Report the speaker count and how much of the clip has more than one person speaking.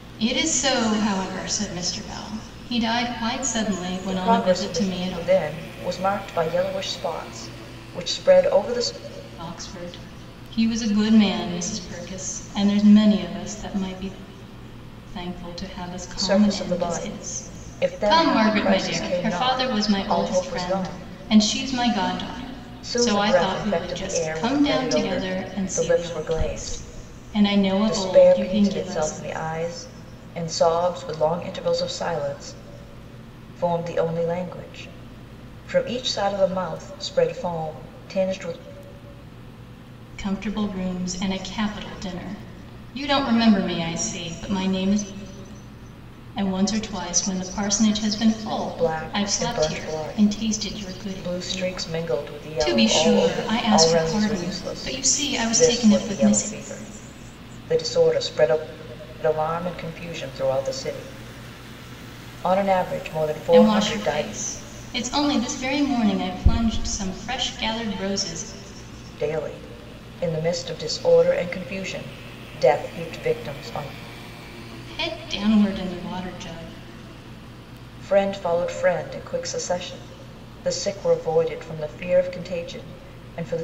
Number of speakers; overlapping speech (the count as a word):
two, about 24%